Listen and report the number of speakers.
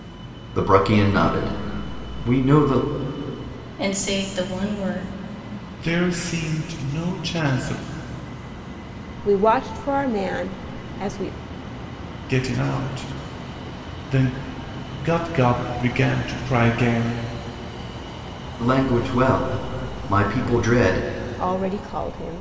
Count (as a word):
four